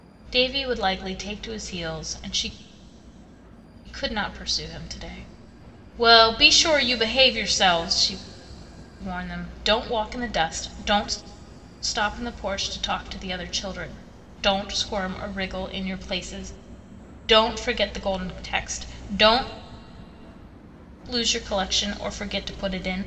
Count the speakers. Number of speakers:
1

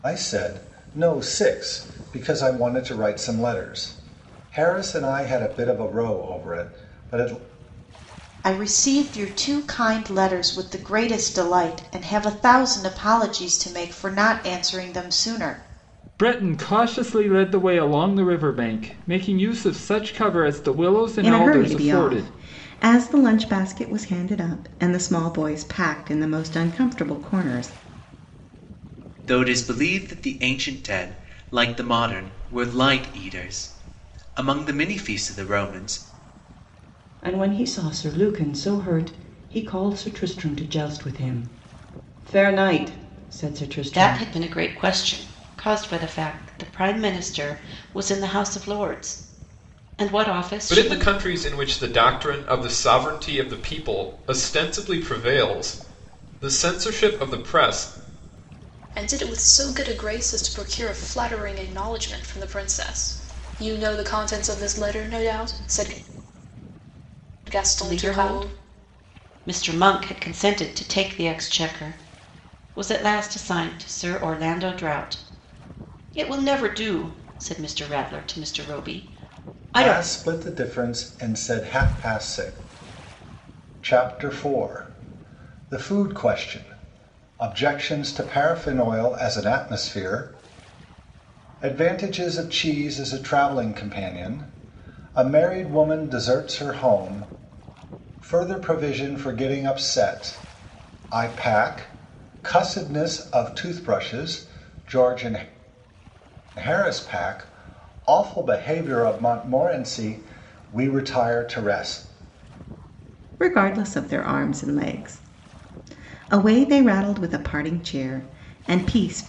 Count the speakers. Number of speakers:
9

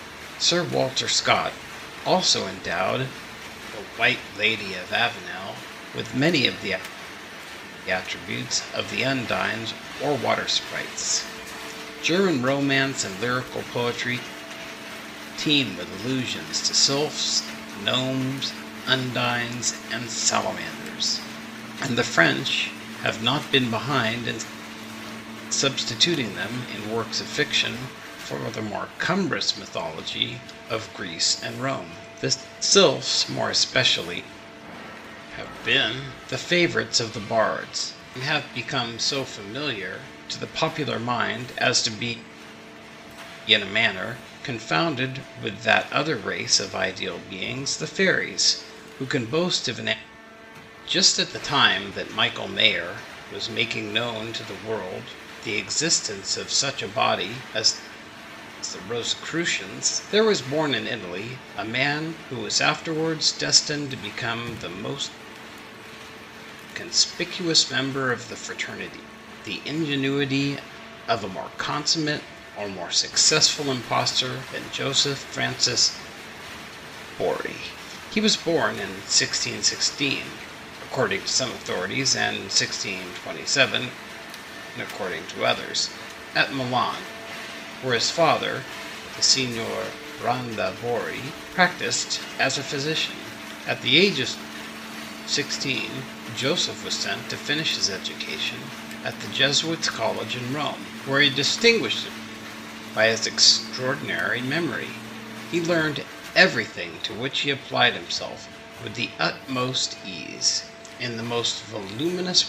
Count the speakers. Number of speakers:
1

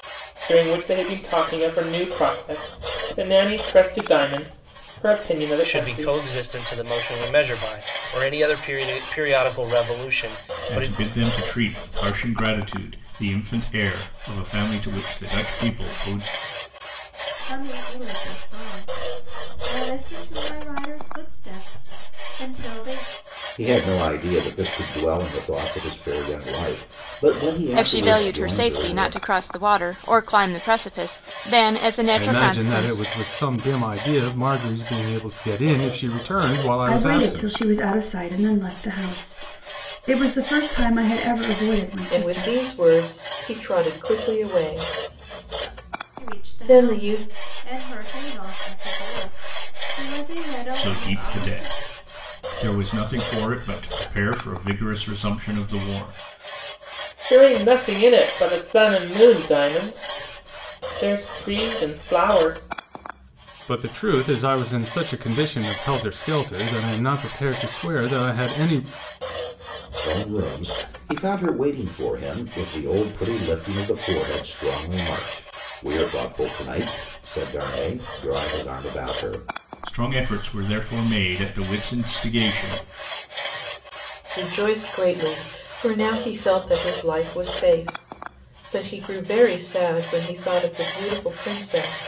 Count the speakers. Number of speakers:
9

